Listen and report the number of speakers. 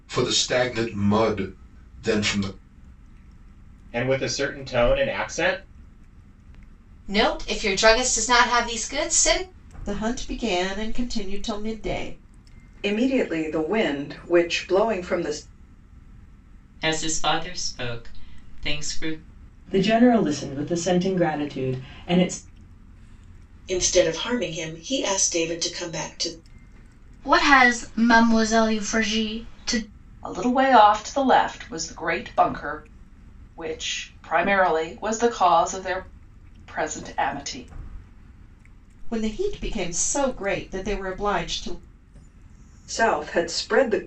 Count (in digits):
10